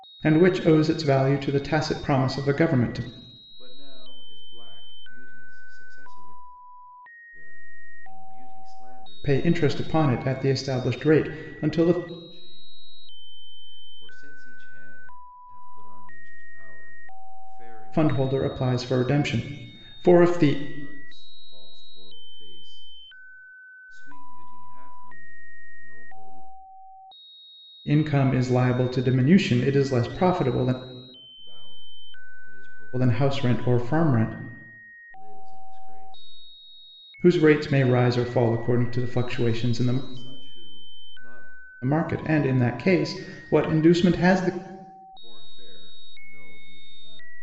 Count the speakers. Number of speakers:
2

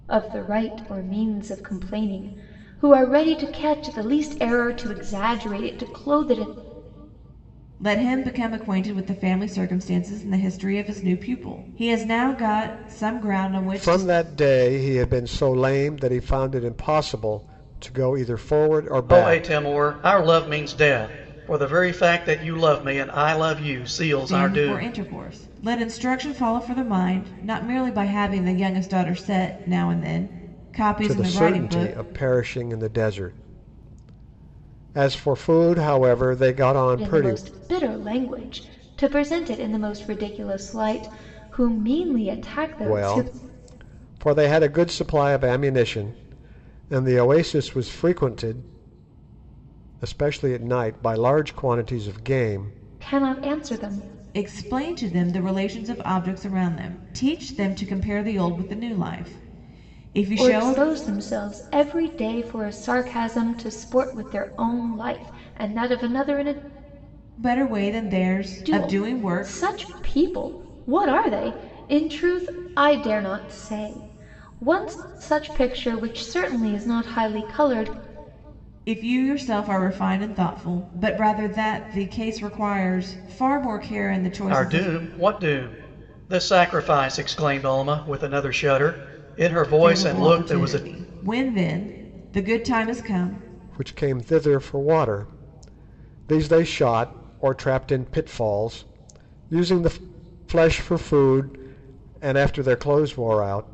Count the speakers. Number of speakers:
4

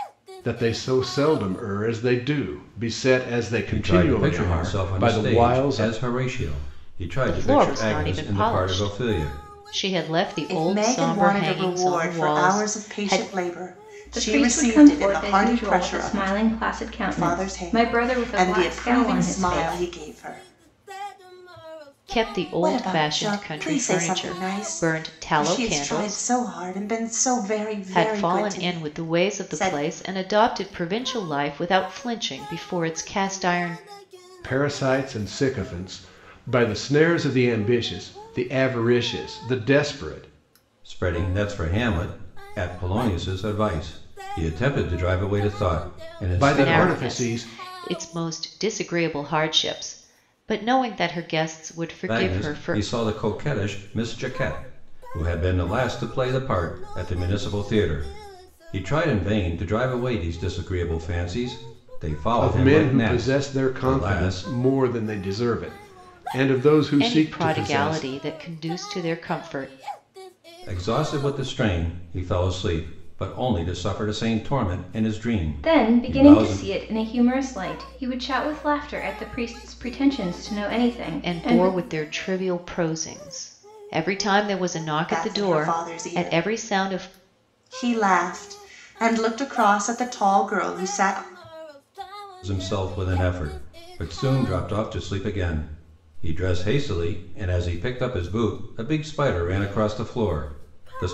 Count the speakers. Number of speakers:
5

